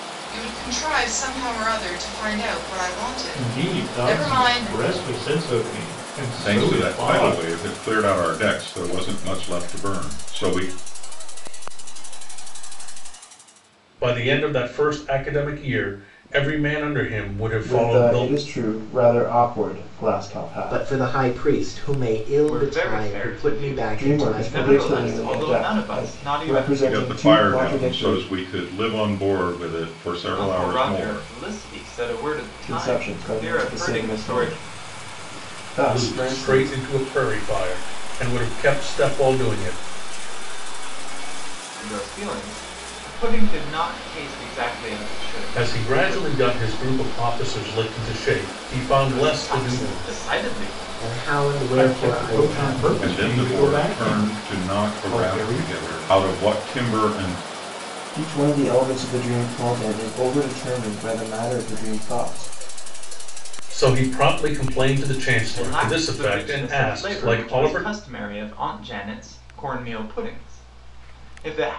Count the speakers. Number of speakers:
8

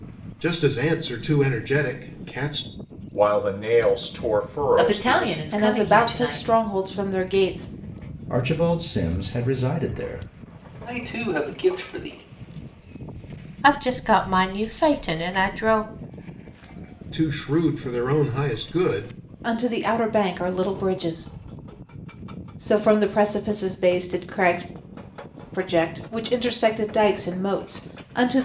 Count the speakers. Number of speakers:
7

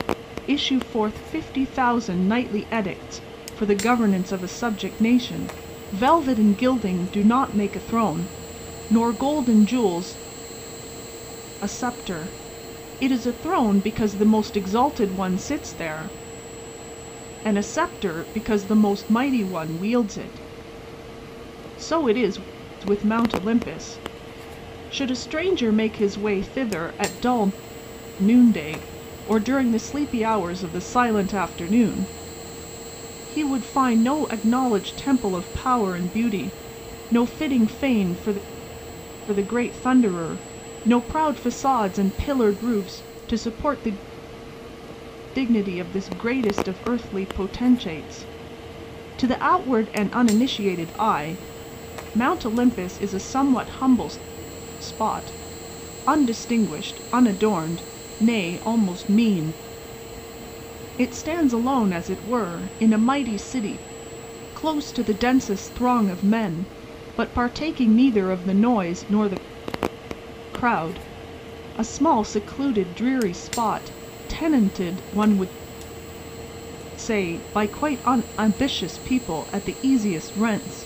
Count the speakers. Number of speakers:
1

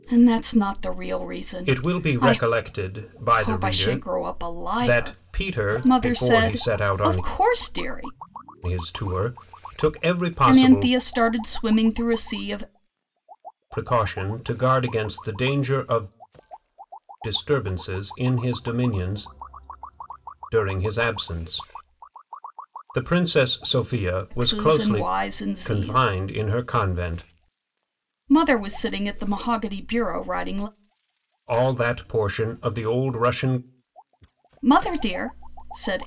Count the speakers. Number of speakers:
2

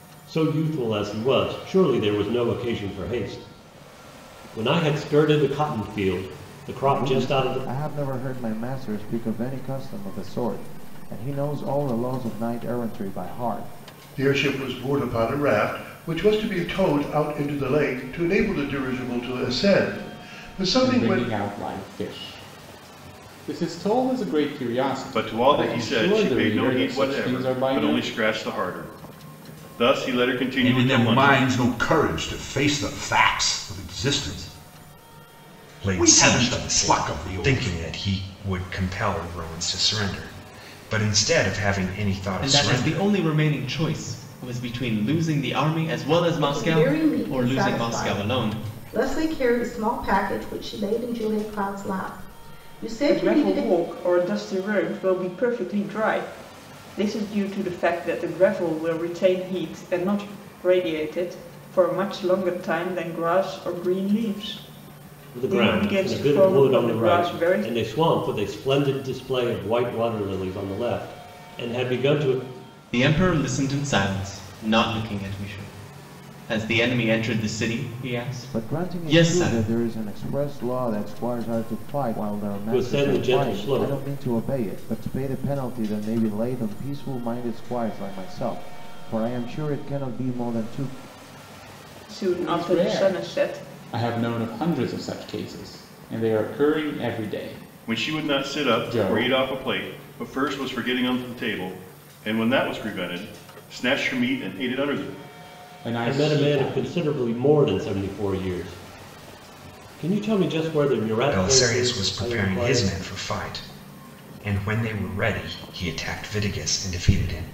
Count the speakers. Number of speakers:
10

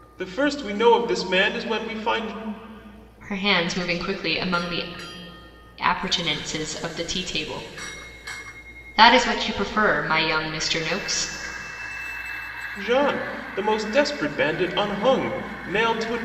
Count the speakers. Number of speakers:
2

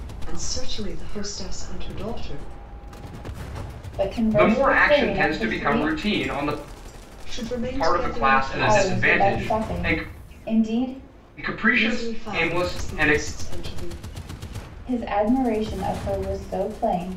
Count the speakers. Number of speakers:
3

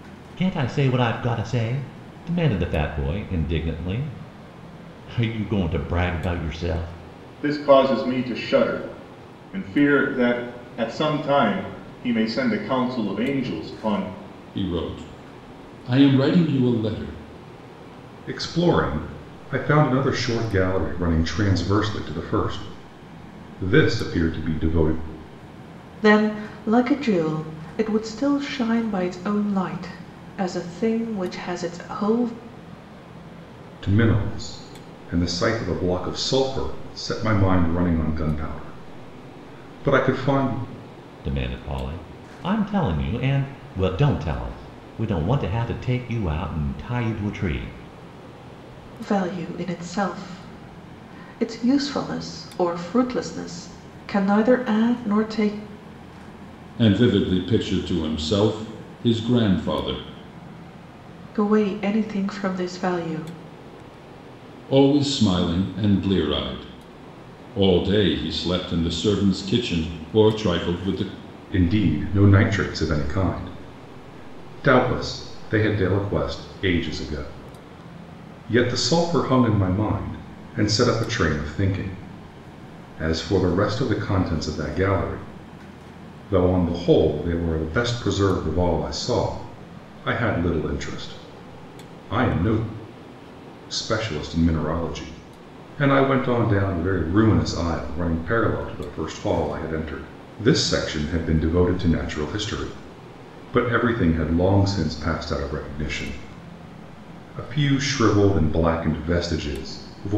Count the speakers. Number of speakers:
5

